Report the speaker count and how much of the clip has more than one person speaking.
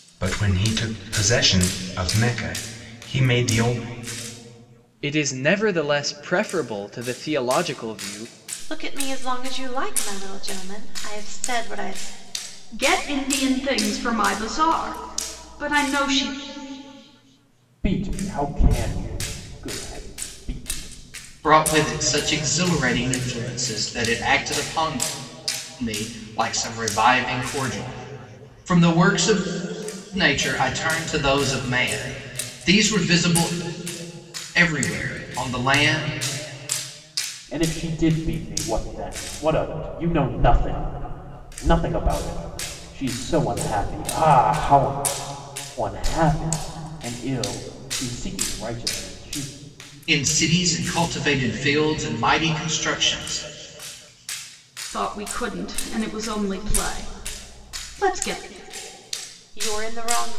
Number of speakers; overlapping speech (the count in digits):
6, no overlap